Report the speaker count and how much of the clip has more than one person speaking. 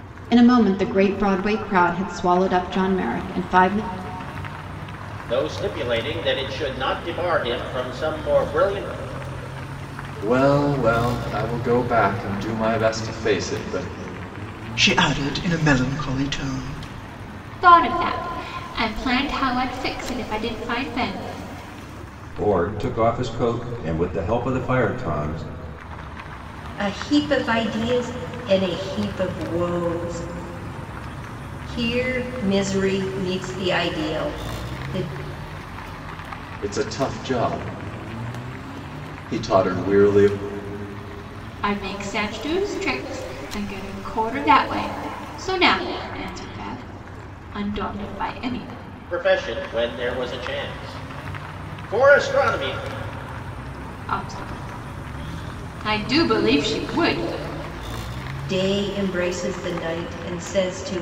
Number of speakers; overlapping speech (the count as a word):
seven, no overlap